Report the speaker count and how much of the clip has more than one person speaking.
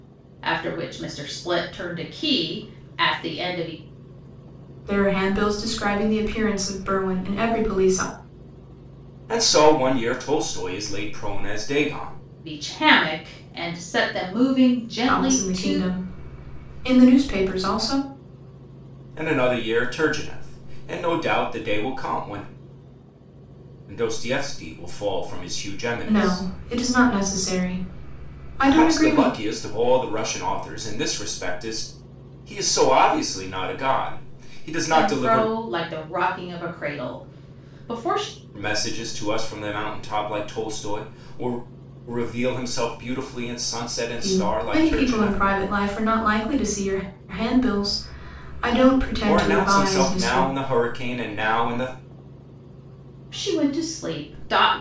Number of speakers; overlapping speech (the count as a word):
three, about 9%